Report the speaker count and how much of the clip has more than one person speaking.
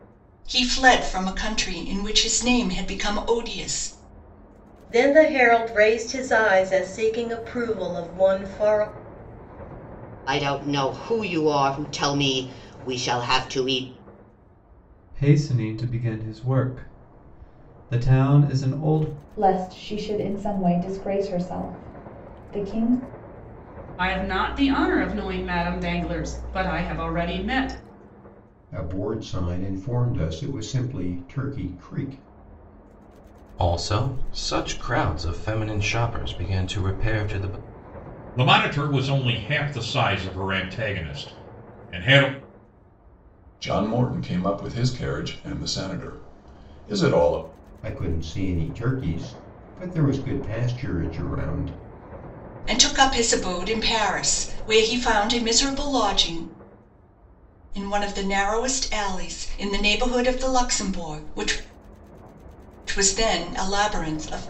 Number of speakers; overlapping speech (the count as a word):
ten, no overlap